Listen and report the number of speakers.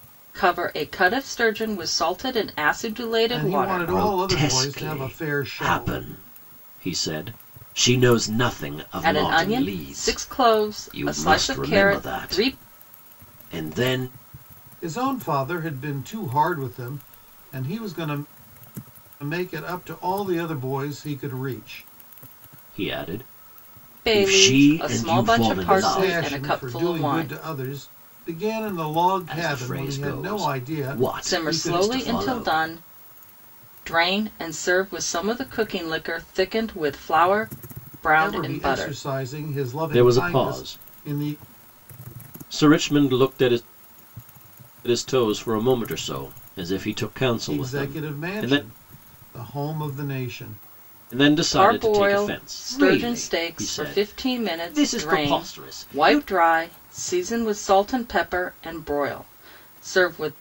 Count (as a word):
three